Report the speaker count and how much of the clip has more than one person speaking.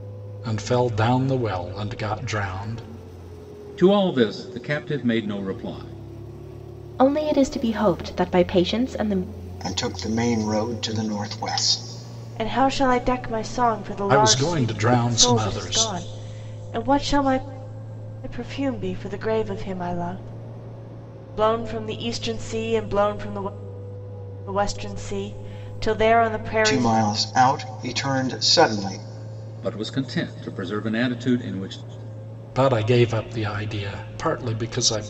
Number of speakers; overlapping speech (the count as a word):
five, about 5%